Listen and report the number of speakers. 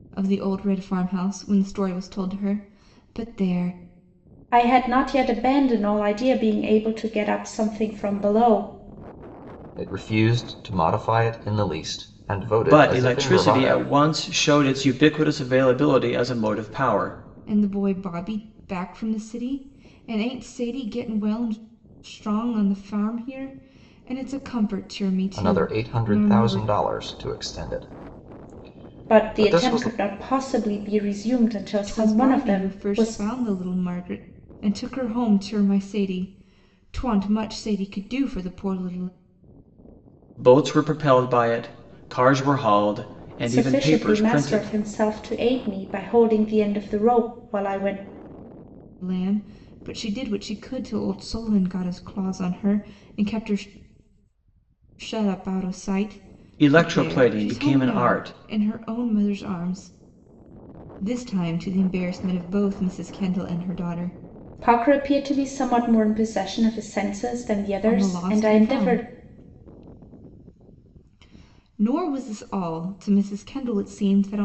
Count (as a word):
four